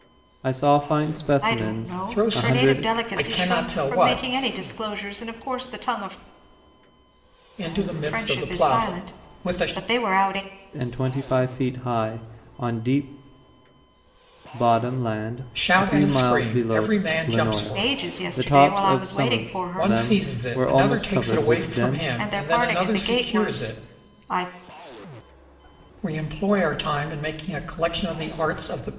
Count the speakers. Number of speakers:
3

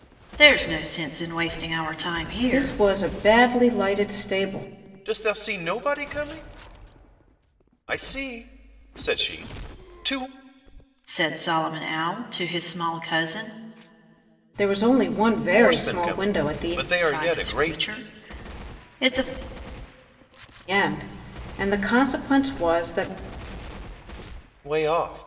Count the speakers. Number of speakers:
3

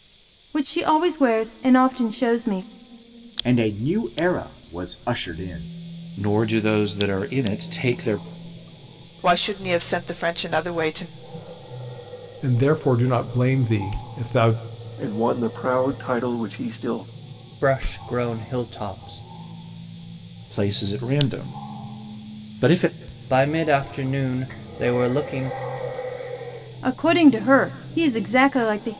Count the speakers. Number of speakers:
7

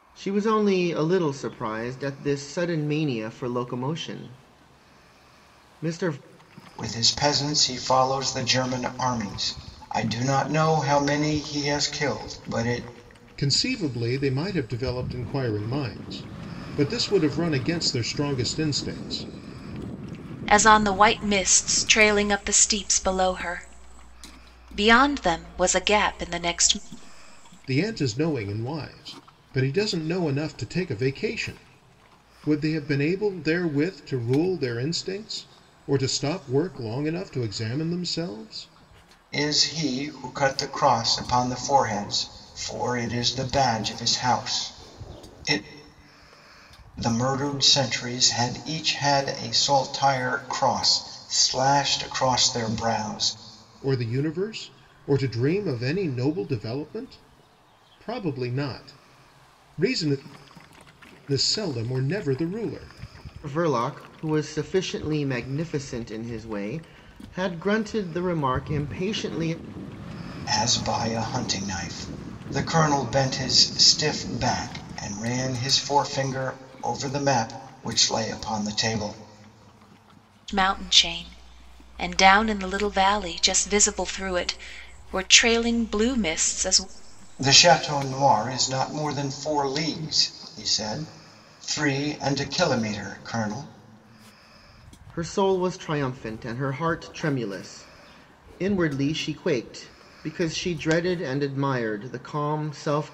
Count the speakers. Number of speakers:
4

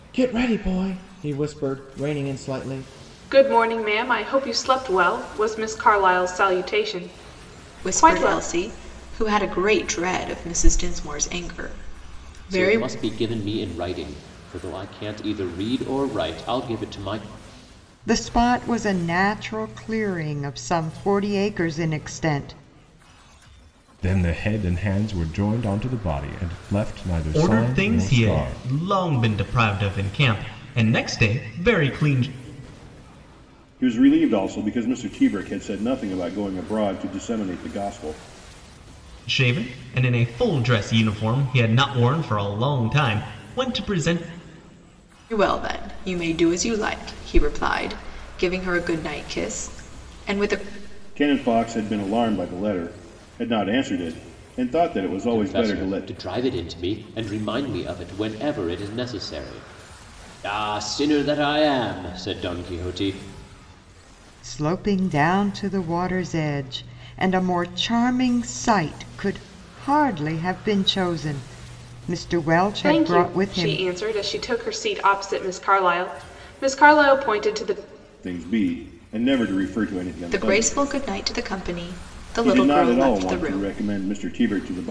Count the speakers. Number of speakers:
8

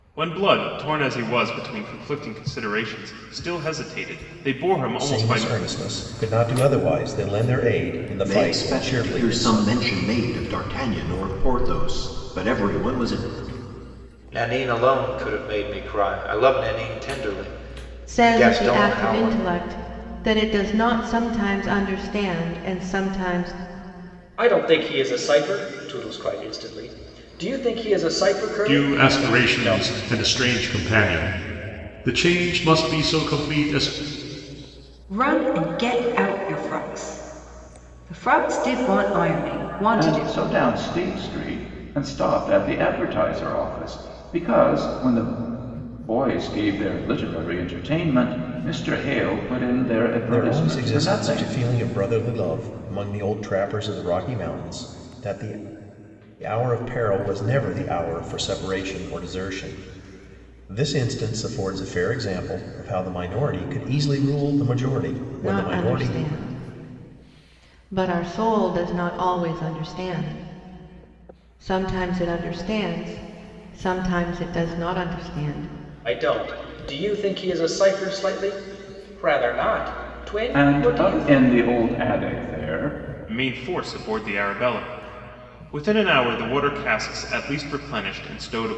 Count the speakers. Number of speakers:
9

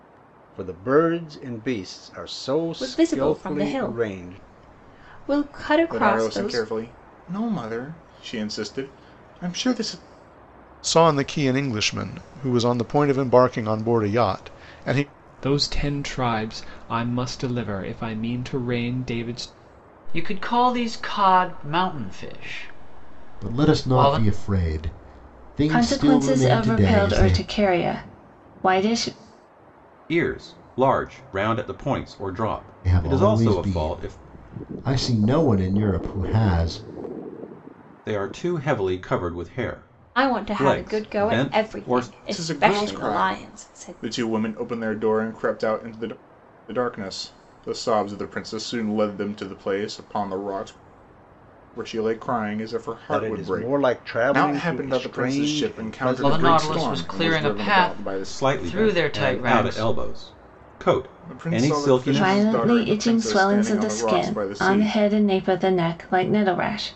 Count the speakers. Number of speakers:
9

